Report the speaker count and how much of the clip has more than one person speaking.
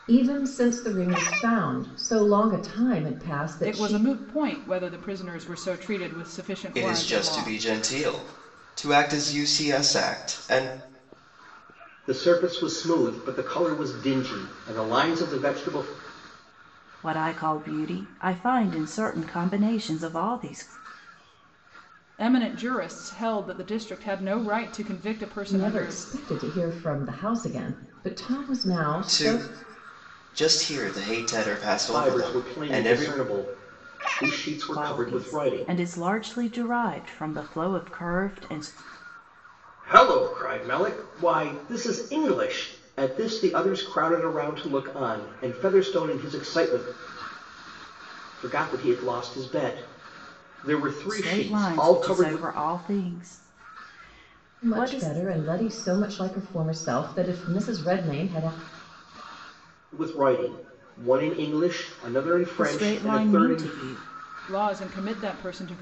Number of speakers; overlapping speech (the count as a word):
five, about 12%